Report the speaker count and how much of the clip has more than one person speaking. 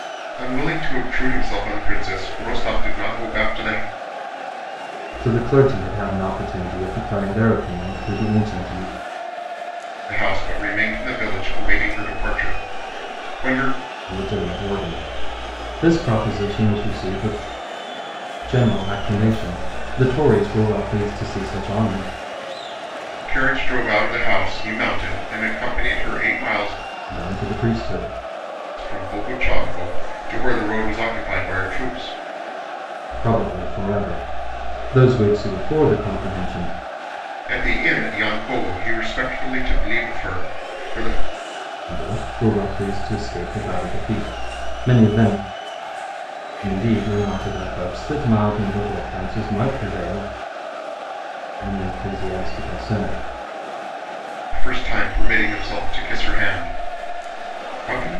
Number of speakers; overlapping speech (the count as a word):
two, no overlap